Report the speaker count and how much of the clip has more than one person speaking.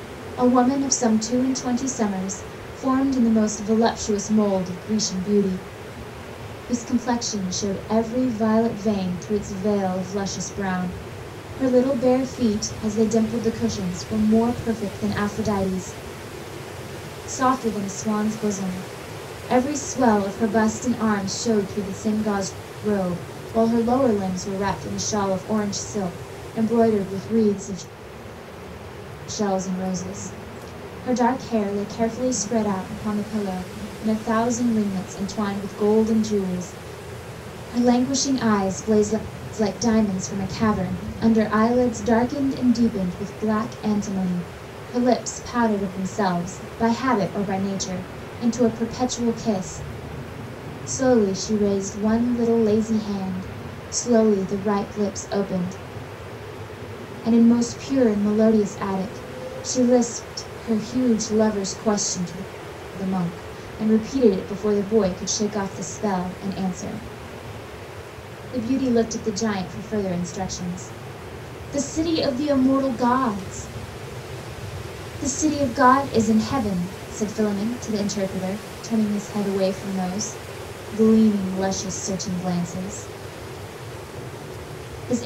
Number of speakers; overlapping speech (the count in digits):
1, no overlap